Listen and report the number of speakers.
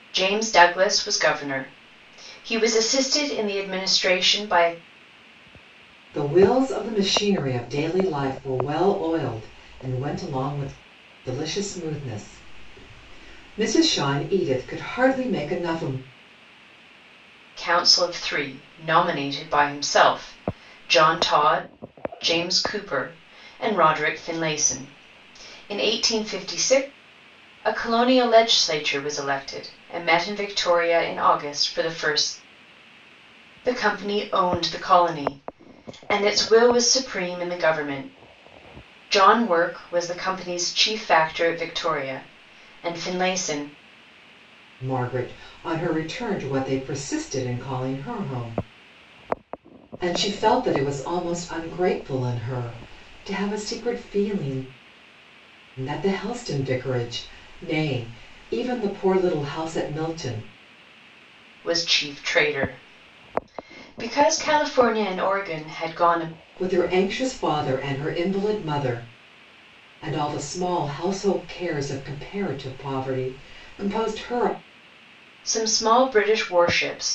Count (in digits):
2